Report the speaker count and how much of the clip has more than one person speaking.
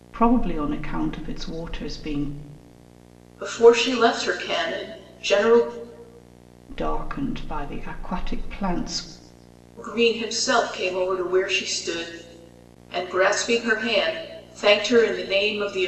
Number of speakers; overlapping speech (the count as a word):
two, no overlap